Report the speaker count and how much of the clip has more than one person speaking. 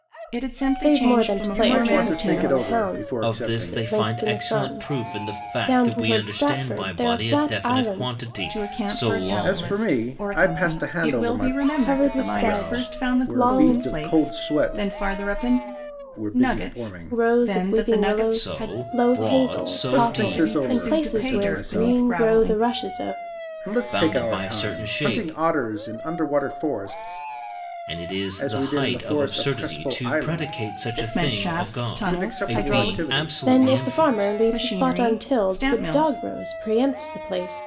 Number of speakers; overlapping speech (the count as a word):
four, about 77%